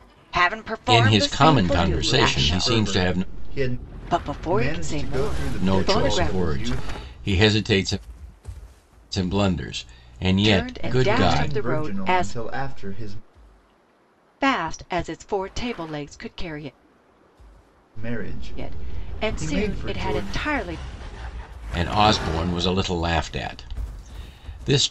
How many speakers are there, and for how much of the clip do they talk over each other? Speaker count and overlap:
3, about 35%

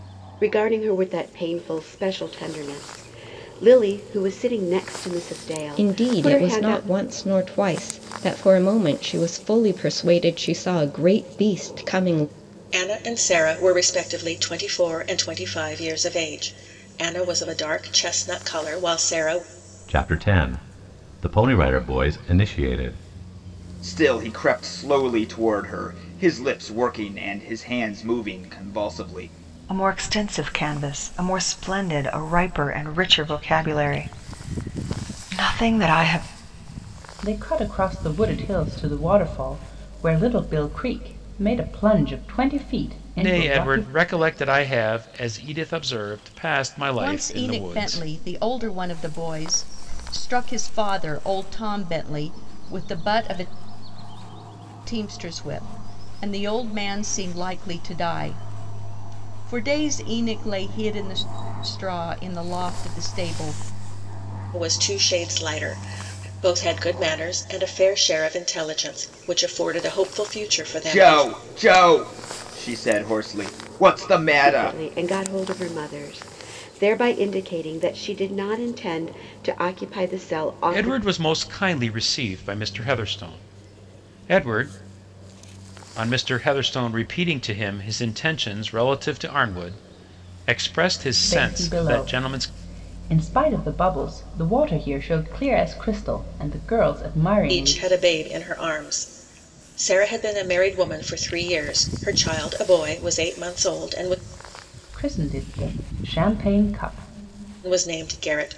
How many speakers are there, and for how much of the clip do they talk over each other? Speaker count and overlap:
9, about 5%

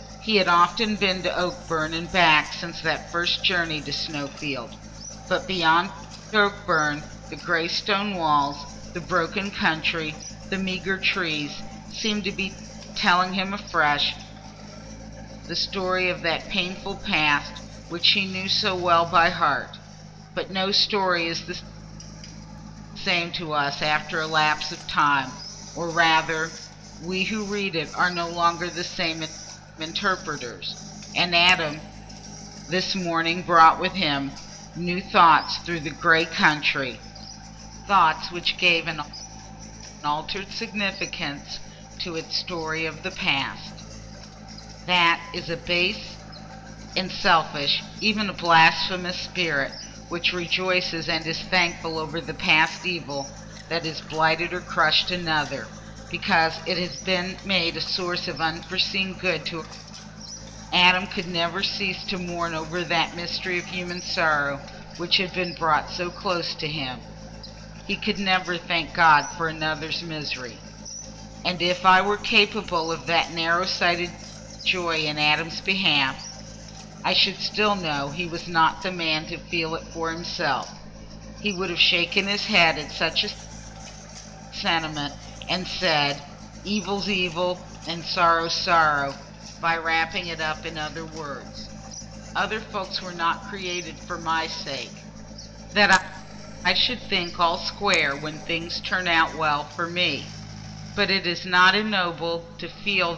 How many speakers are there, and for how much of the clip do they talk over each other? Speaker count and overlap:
1, no overlap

